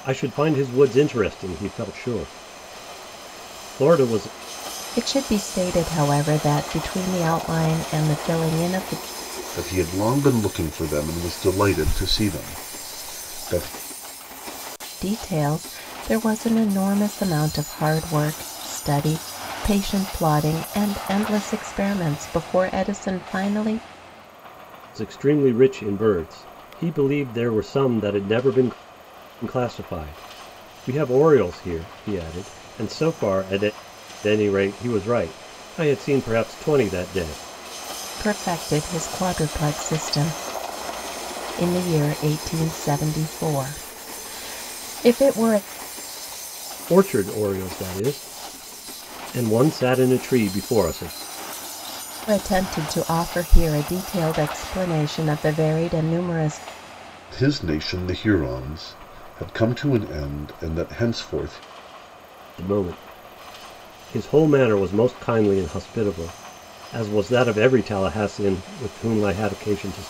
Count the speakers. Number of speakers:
3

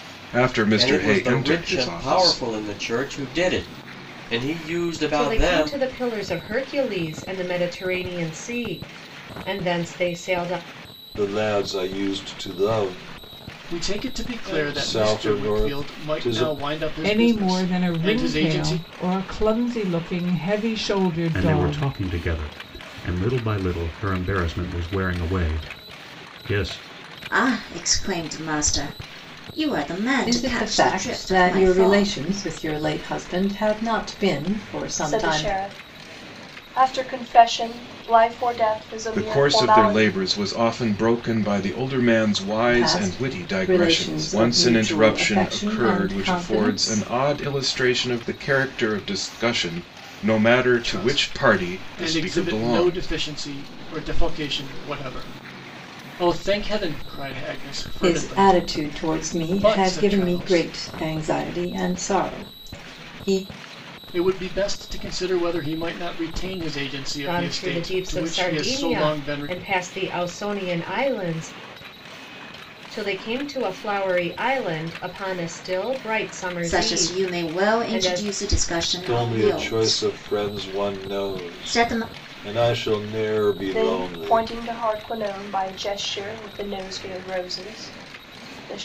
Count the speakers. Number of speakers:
10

